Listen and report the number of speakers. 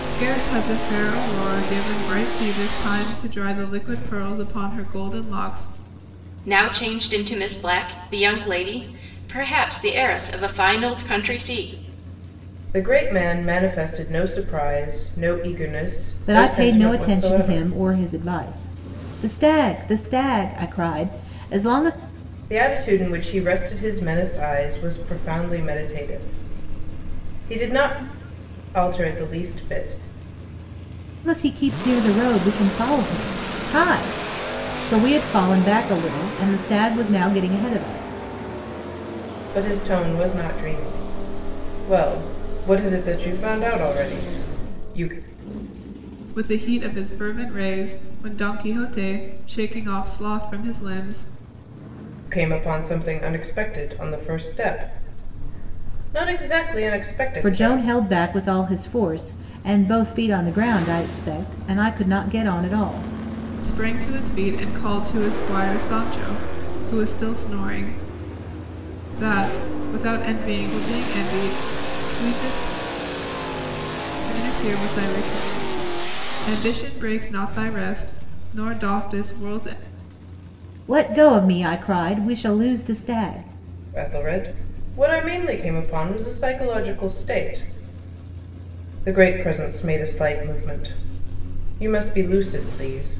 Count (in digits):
4